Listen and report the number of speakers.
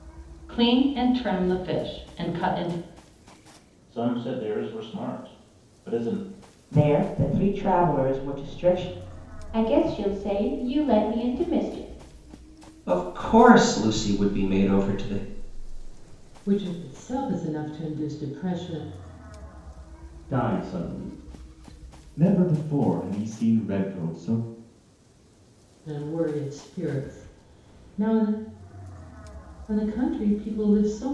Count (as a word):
eight